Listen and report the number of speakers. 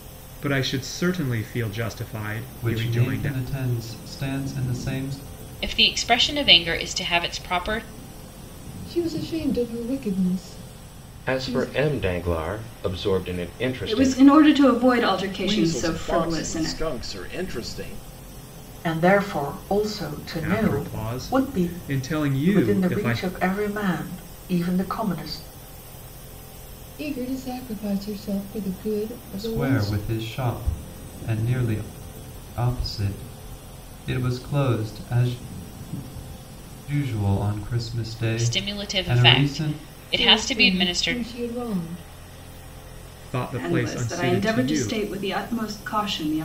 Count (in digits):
8